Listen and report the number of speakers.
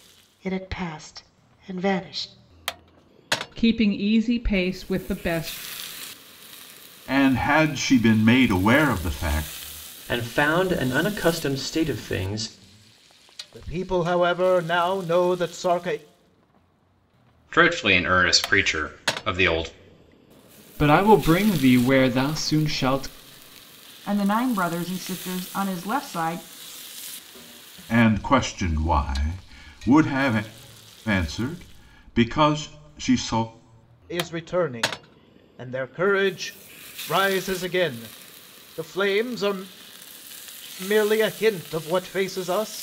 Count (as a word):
eight